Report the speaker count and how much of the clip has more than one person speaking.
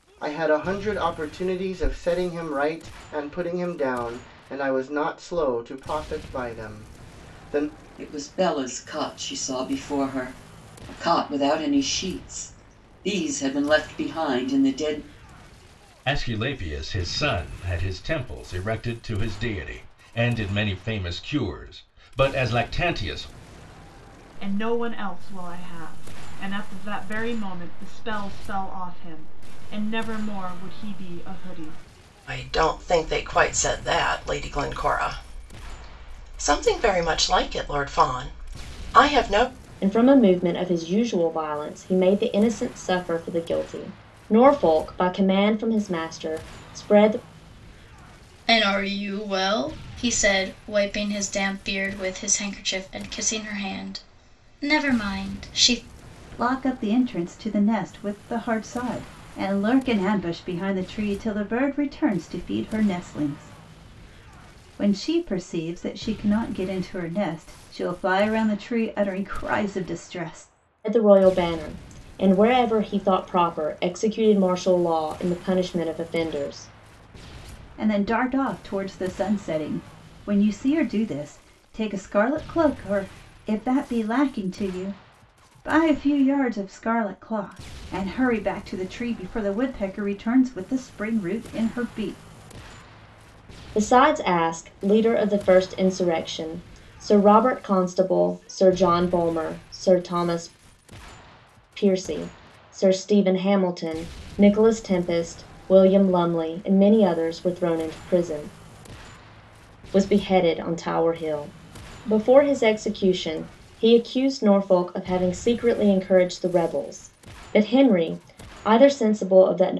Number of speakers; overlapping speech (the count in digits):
8, no overlap